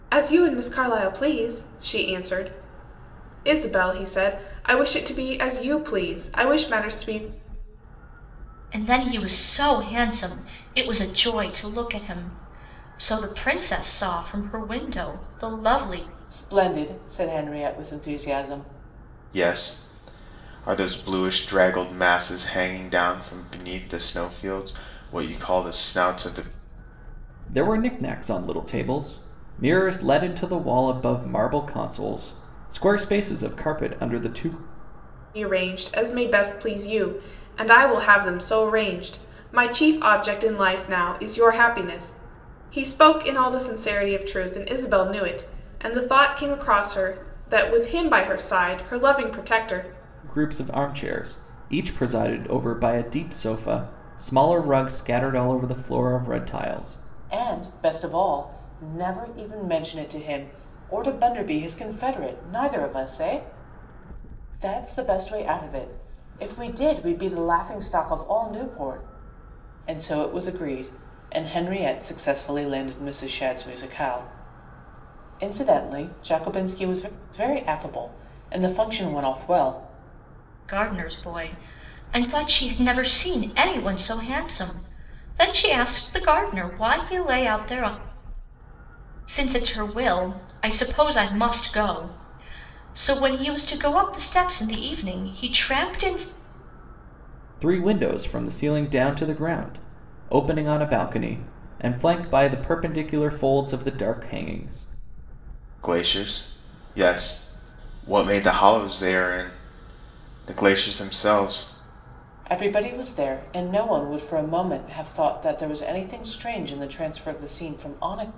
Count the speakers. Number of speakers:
five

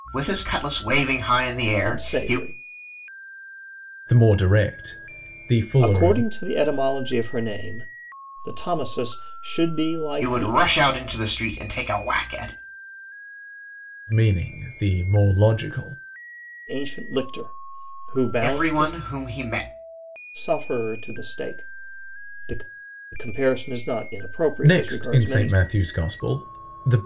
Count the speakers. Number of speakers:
three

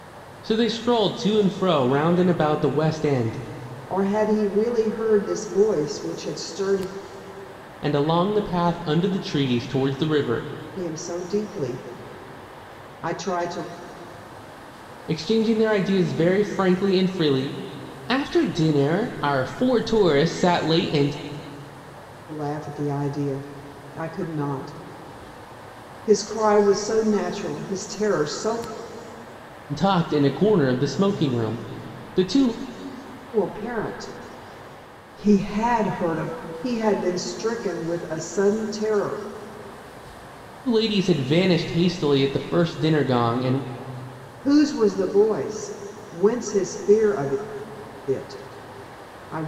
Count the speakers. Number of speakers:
two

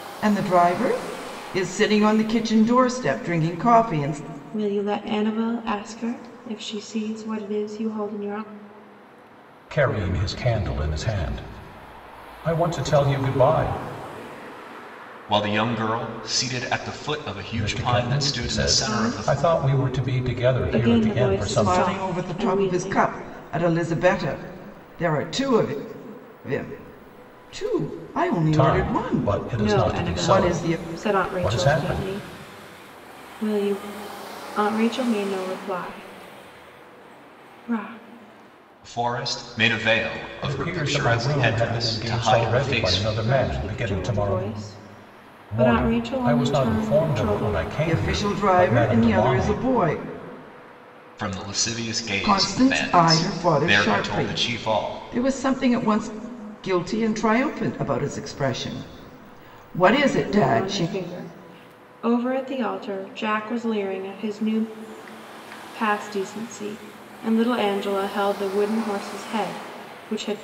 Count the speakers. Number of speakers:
four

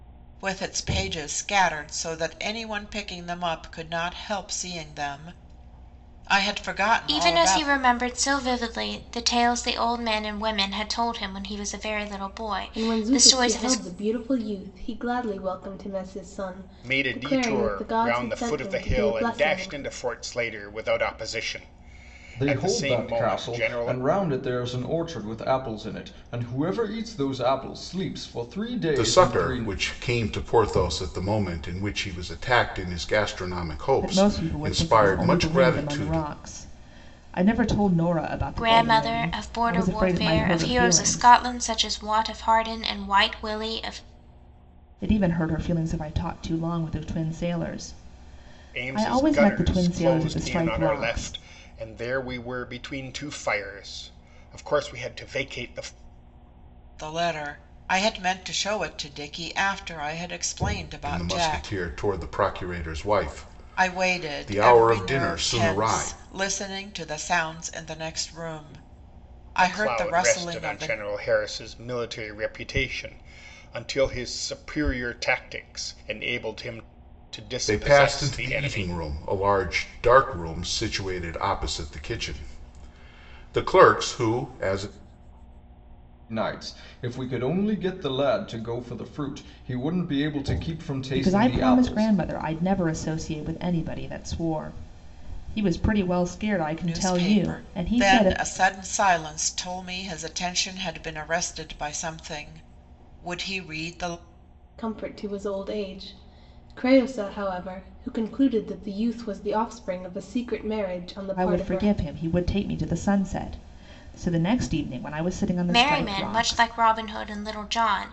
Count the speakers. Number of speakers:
seven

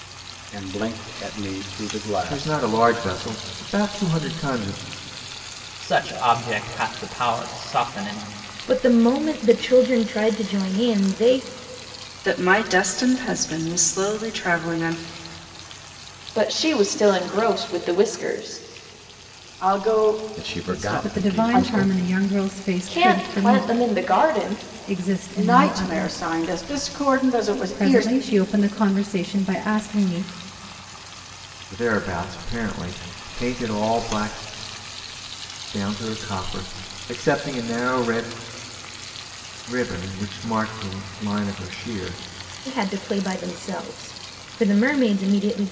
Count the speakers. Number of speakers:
nine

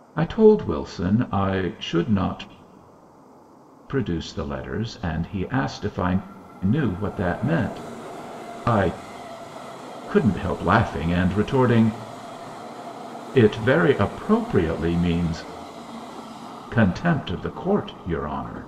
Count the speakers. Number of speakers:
one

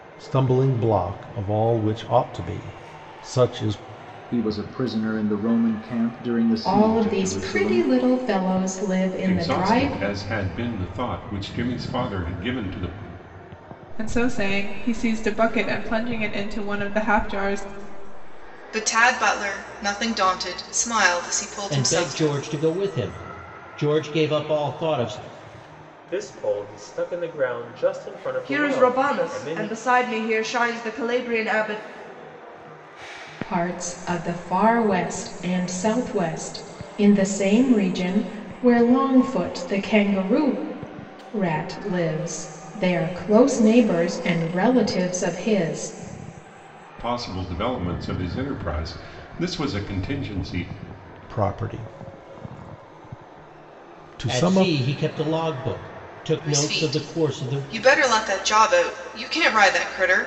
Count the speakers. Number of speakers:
nine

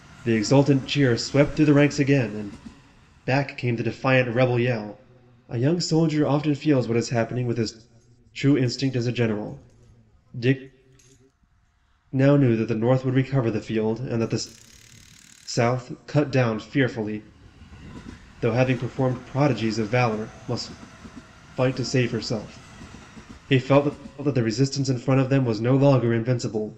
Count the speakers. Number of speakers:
one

